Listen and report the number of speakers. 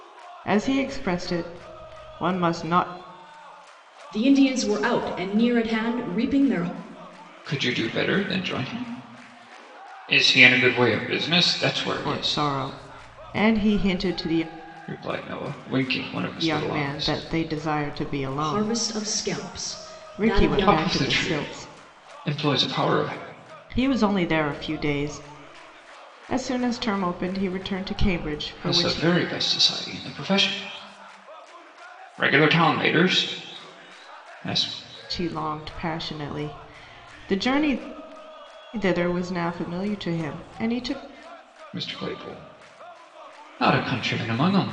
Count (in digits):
3